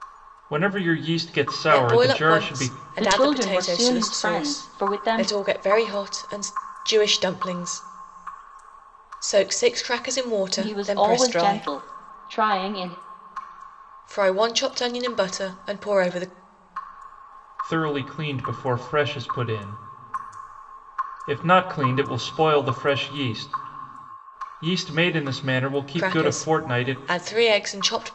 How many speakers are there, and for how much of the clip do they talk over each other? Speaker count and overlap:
3, about 20%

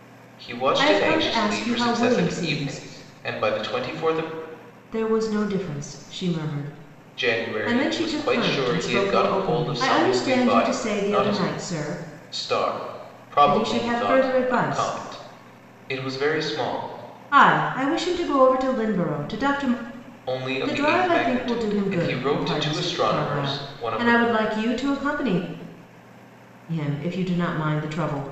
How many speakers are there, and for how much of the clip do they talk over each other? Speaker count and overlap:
2, about 40%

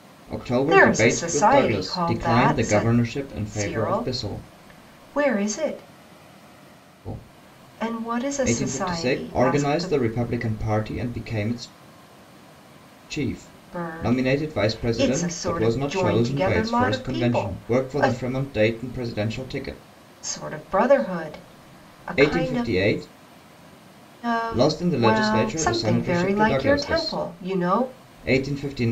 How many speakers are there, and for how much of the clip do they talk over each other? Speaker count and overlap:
2, about 52%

